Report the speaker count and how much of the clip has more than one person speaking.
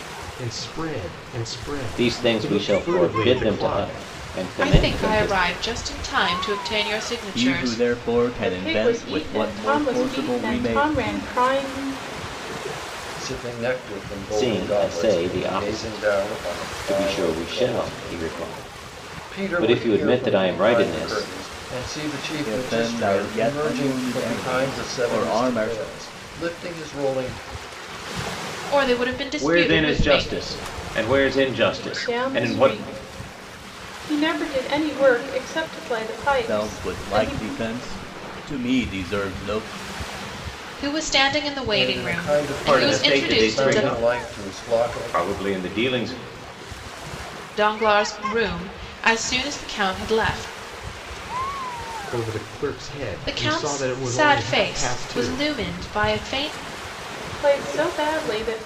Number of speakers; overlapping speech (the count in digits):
6, about 42%